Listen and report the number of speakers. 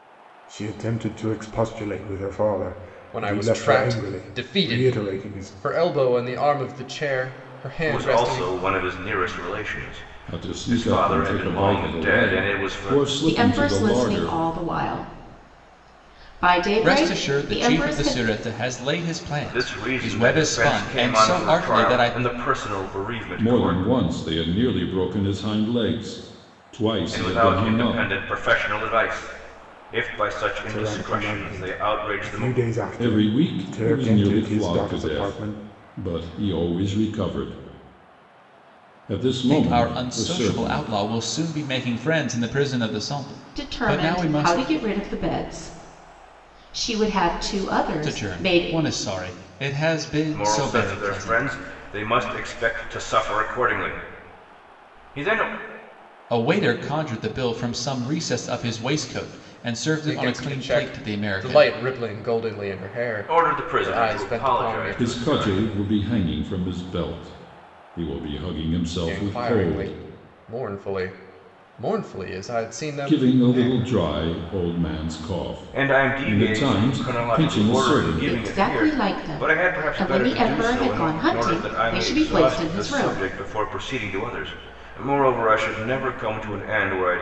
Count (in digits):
6